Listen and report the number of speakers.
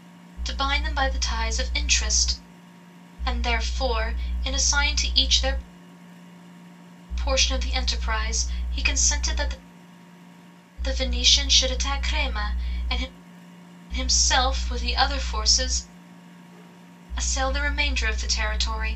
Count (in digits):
1